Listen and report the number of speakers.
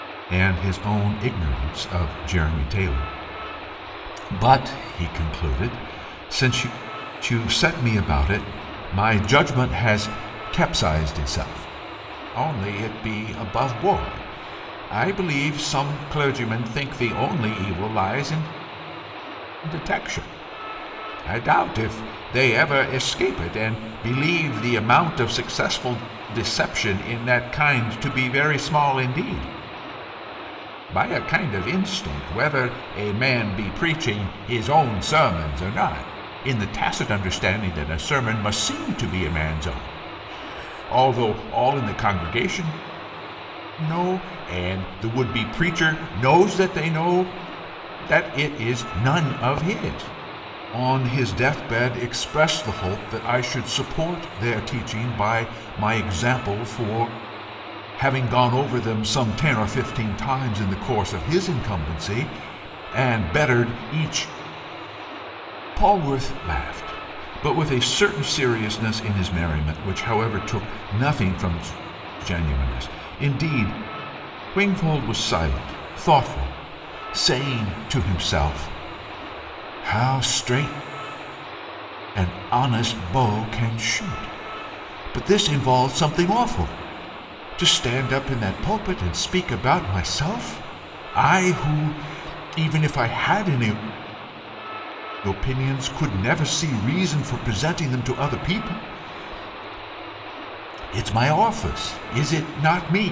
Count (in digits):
1